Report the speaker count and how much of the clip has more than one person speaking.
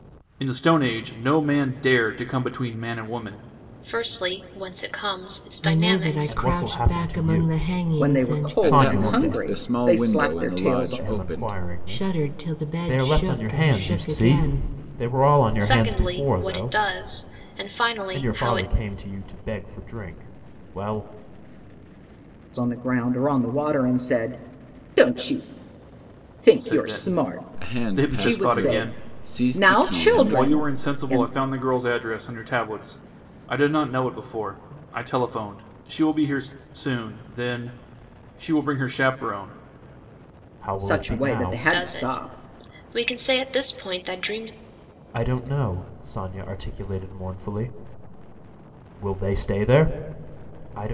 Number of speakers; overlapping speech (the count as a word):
six, about 33%